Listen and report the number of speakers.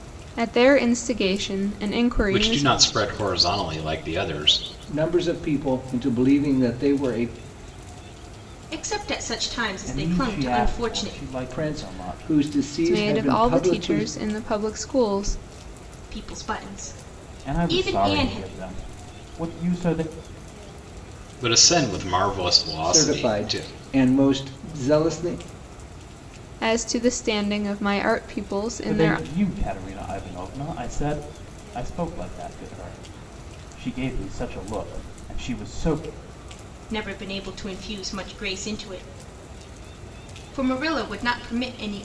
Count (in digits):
5